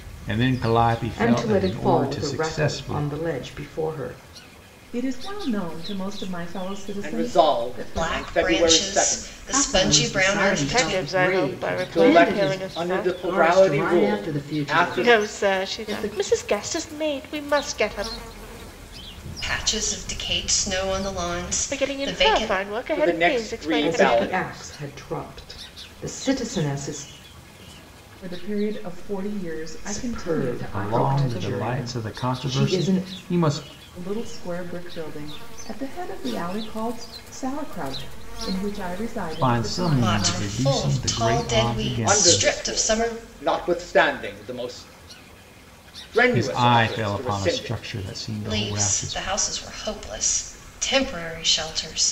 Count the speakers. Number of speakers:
7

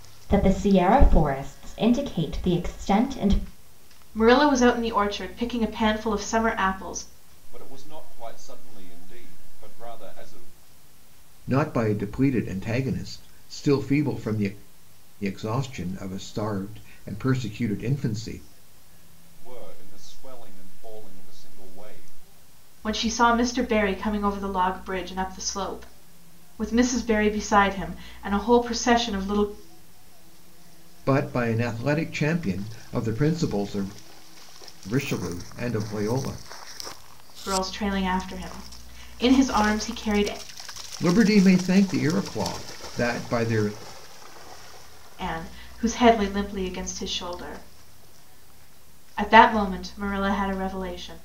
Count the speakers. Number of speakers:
4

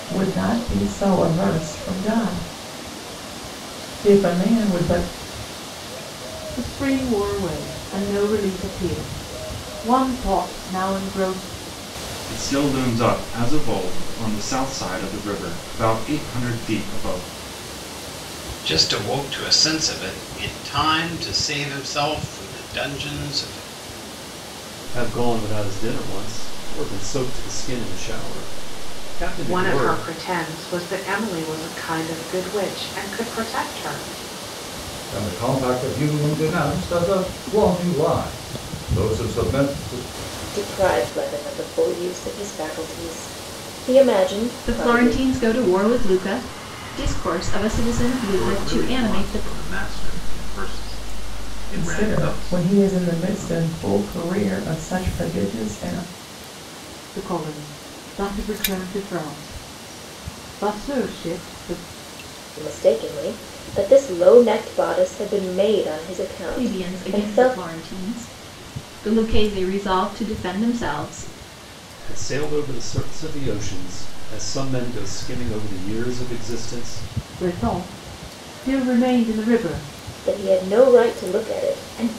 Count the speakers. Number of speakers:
10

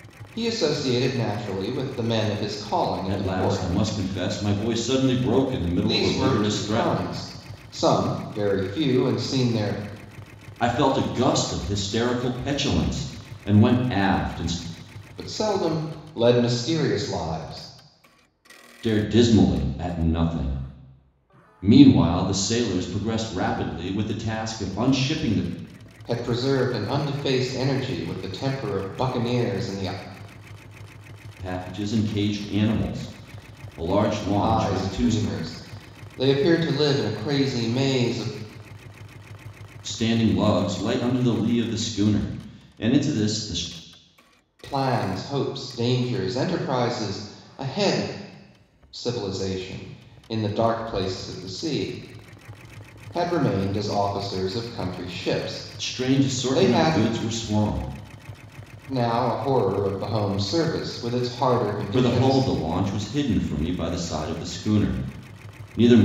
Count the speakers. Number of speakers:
2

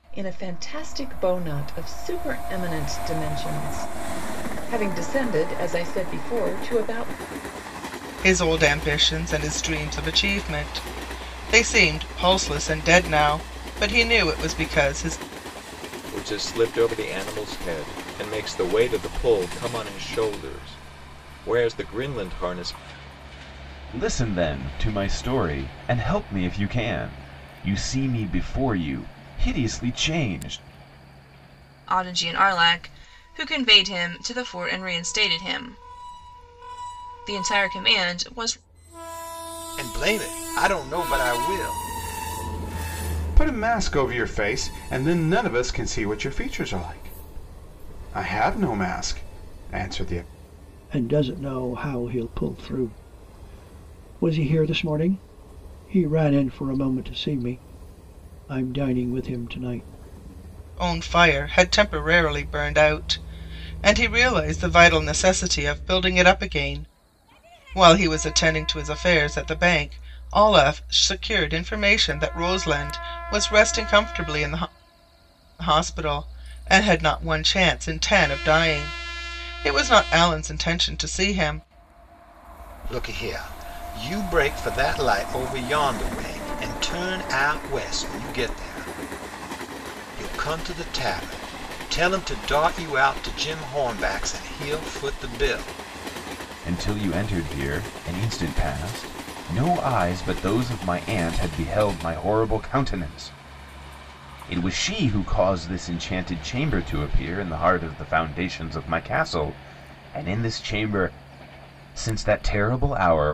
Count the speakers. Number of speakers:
8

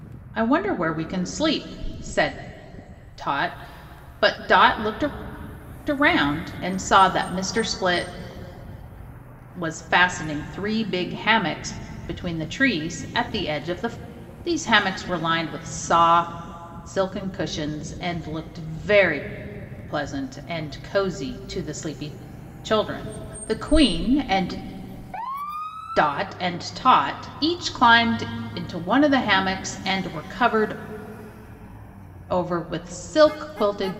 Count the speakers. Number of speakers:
1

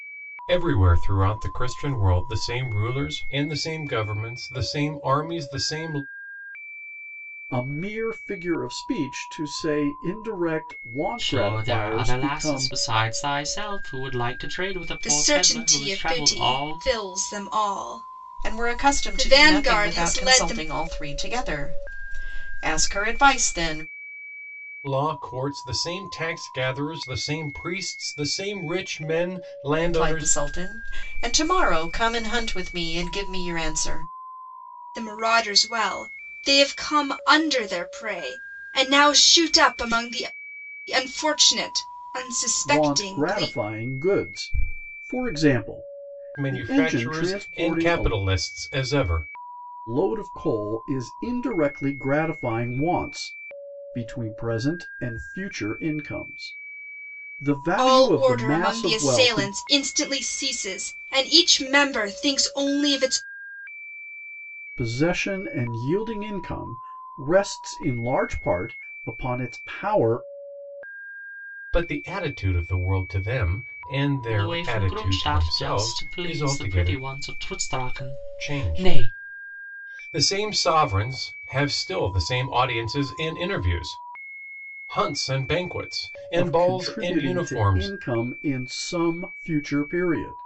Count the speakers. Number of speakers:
5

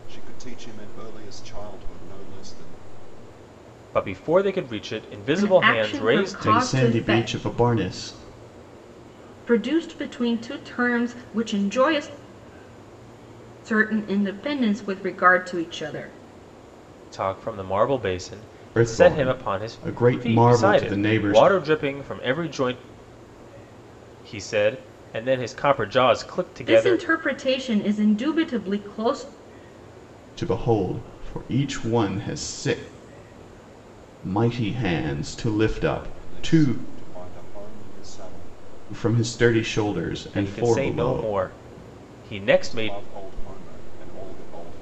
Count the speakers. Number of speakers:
4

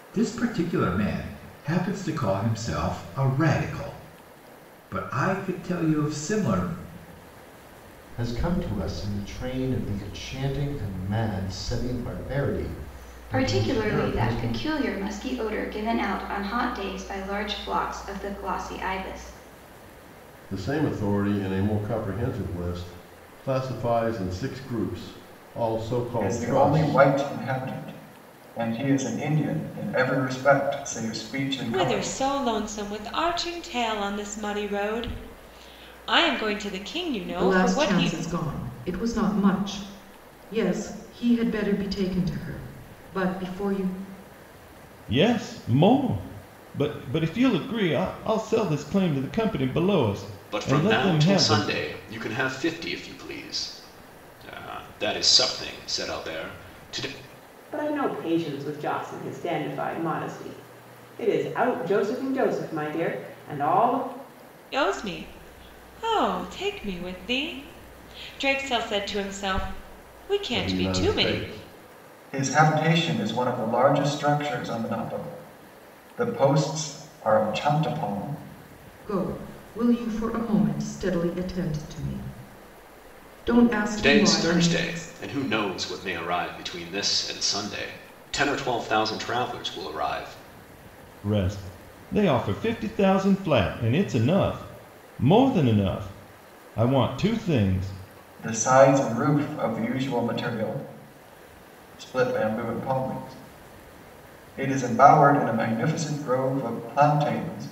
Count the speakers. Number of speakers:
10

